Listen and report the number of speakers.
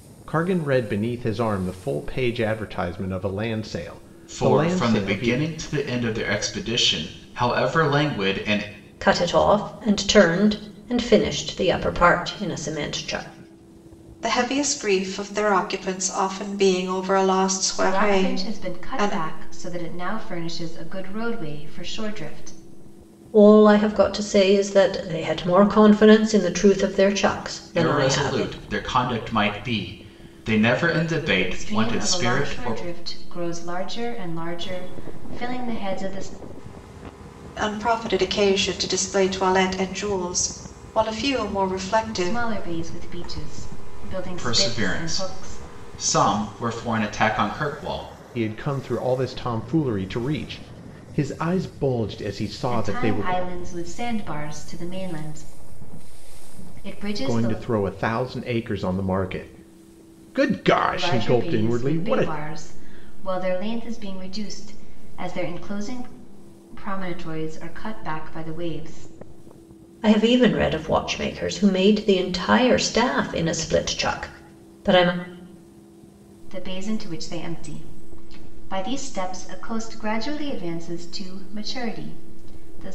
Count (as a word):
five